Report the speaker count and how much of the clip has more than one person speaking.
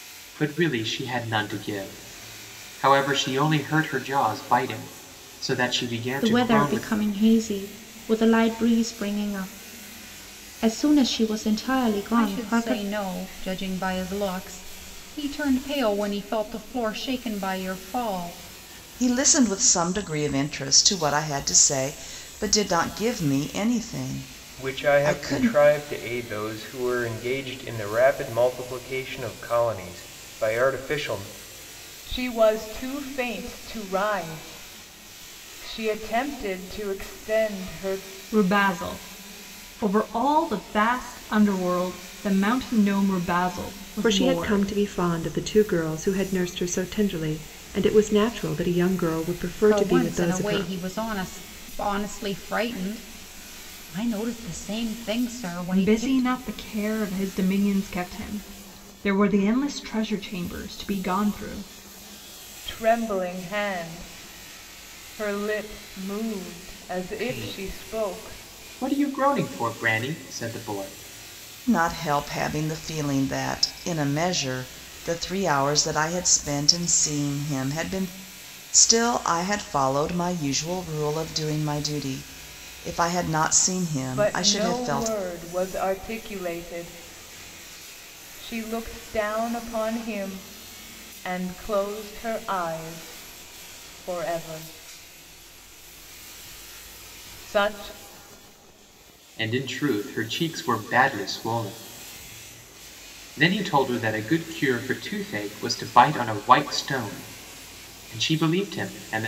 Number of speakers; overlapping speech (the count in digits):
8, about 7%